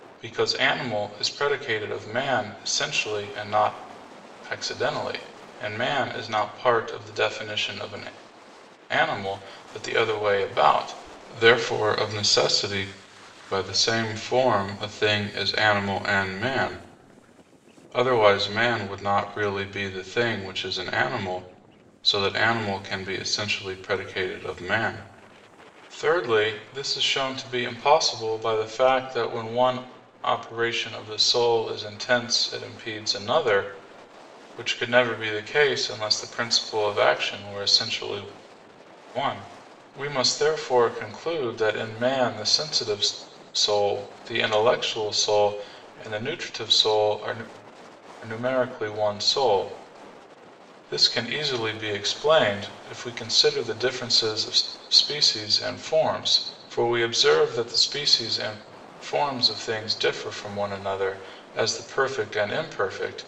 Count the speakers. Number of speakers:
one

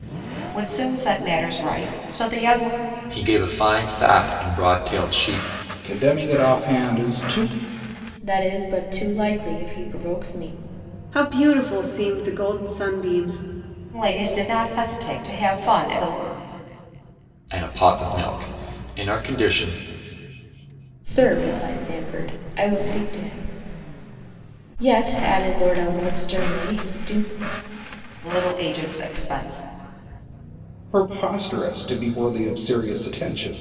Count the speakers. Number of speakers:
five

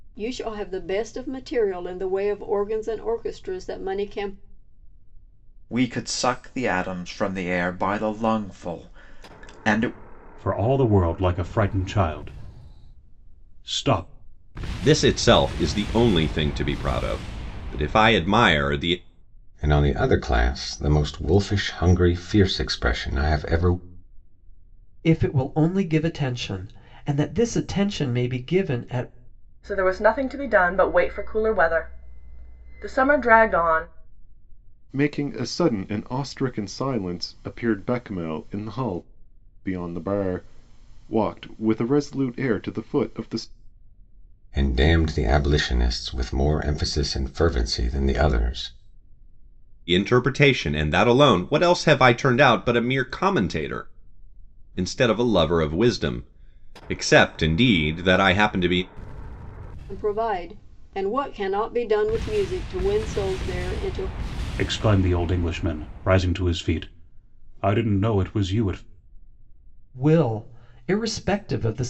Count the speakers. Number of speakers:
eight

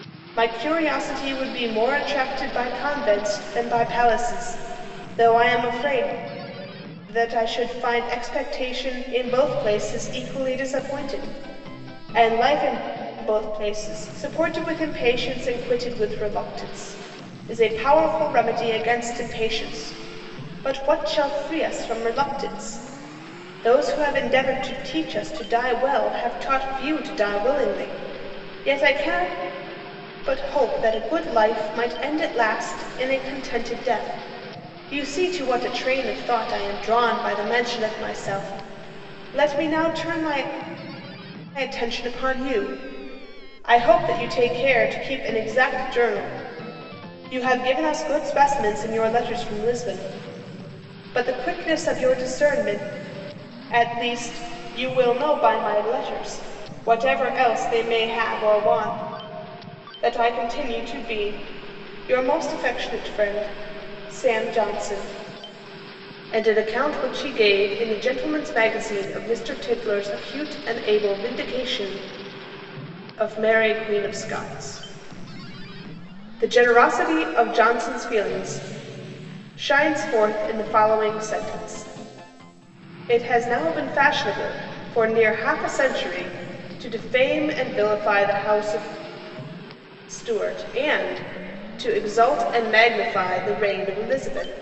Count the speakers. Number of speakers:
one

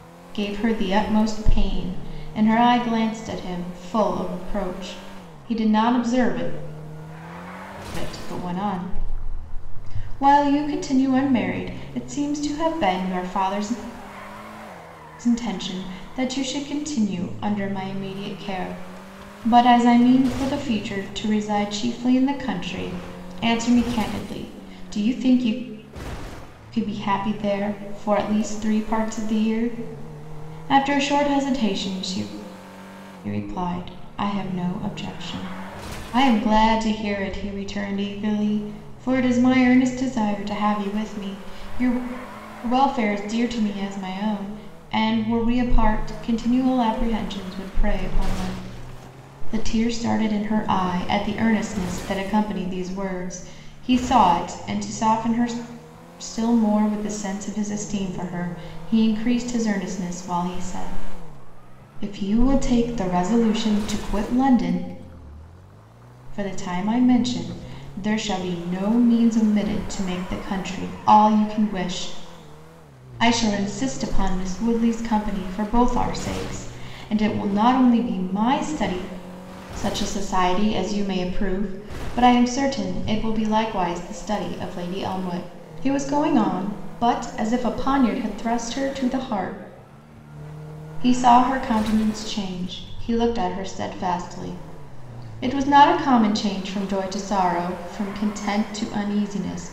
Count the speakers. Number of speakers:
one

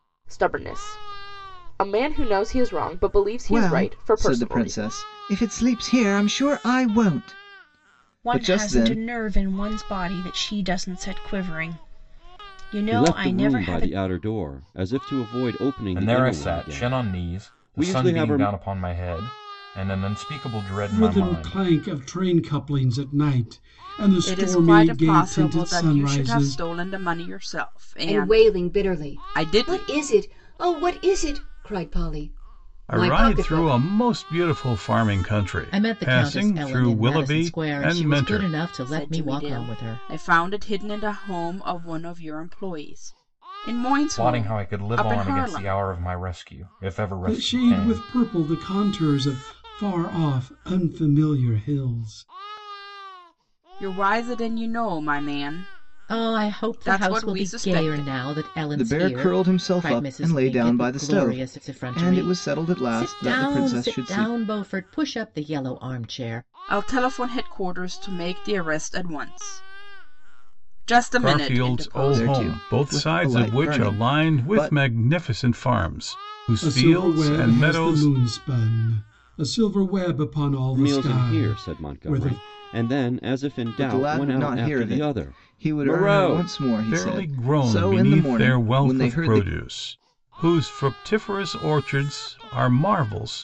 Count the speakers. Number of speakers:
ten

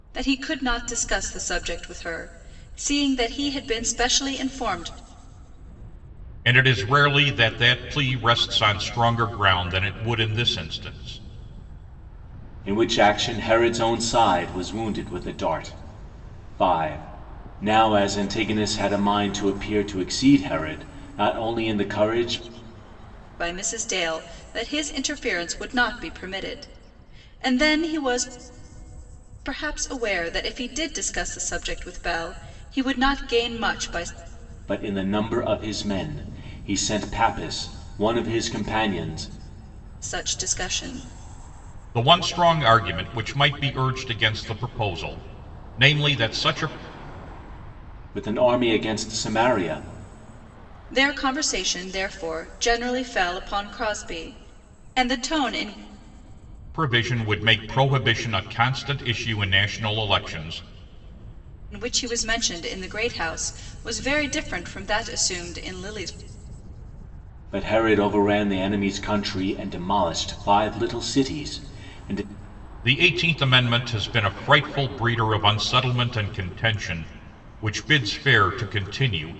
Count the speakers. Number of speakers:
three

